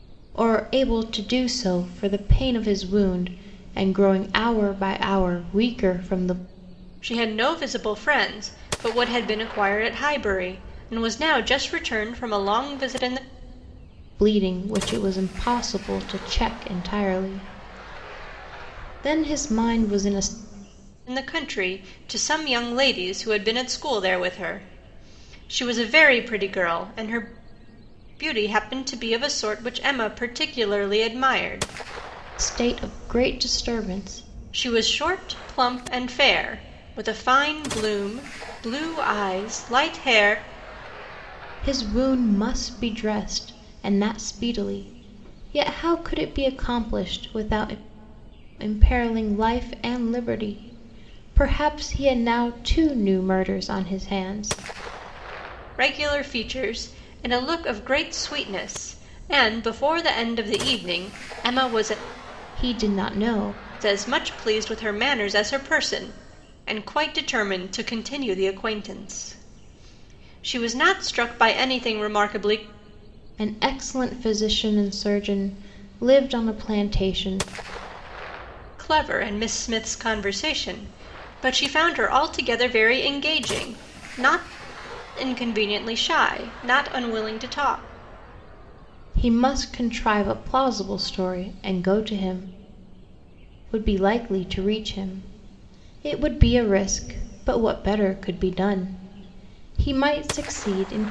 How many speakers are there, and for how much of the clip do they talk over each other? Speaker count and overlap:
2, no overlap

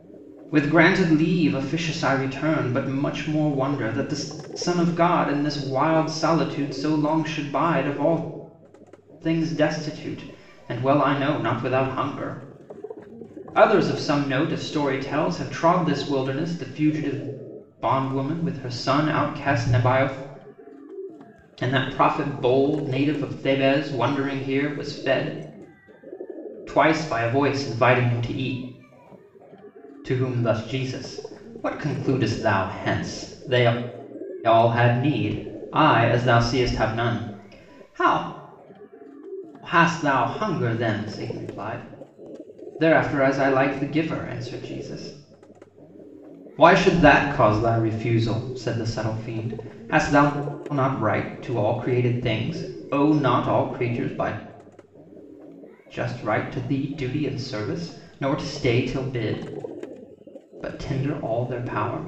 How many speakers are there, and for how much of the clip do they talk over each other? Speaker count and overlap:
1, no overlap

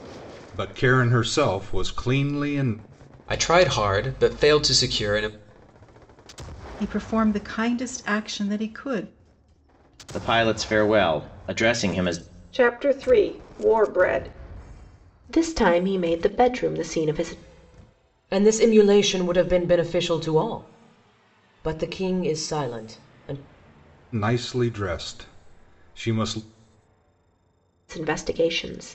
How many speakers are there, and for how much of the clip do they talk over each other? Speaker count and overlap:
7, no overlap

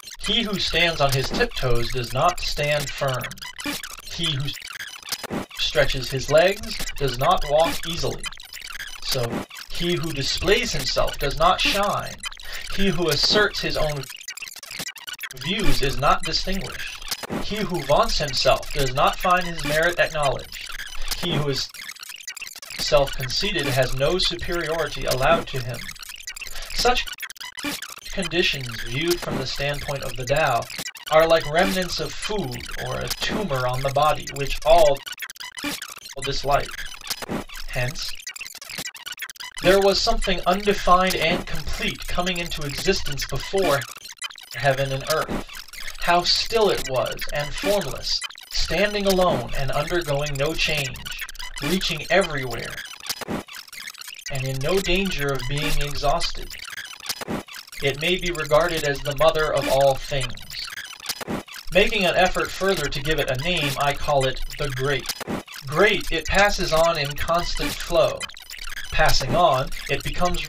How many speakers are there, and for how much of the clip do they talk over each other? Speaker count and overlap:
1, no overlap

